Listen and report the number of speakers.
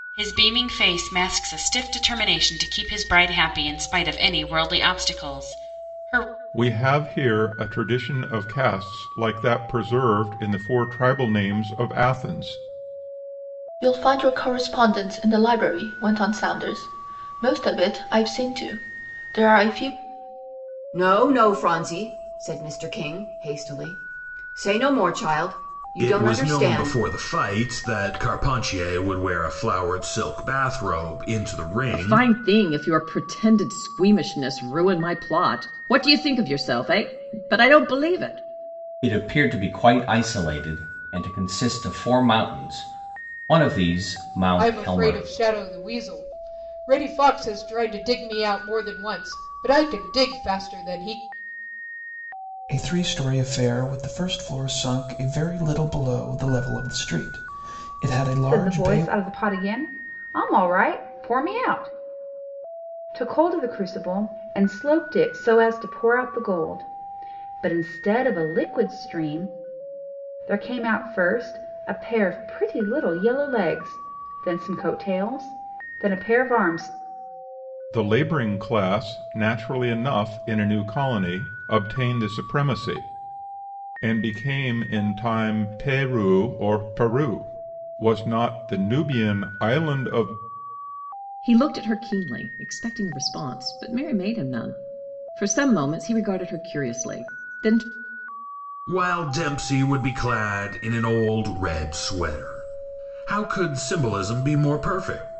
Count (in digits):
10